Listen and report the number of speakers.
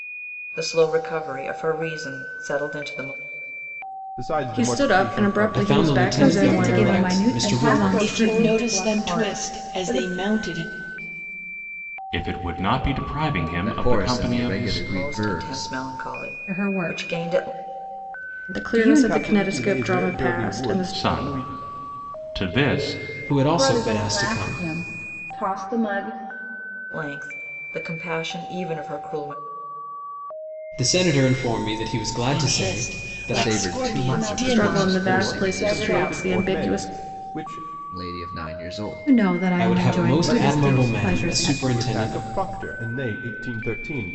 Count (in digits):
9